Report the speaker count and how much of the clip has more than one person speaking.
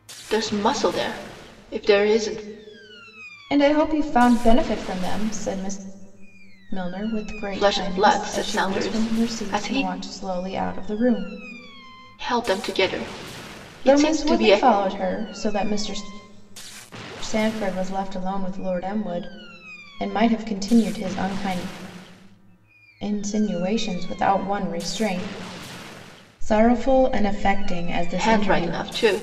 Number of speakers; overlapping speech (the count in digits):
2, about 13%